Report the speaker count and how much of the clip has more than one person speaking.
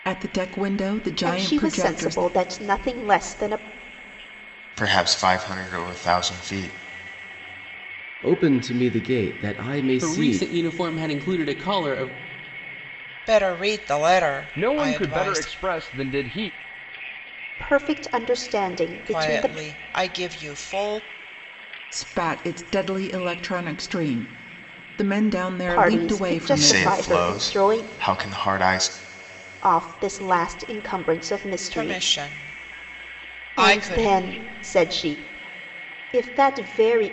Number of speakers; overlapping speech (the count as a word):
seven, about 17%